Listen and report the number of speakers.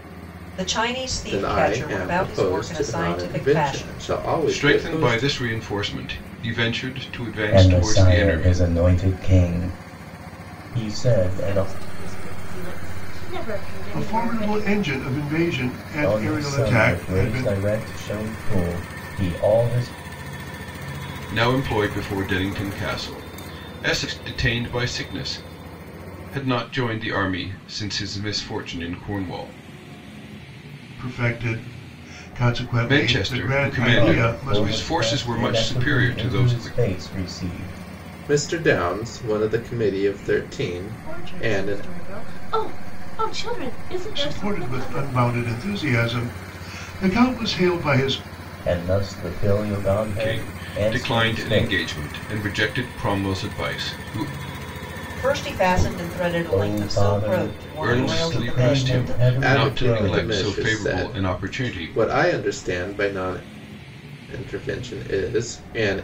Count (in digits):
6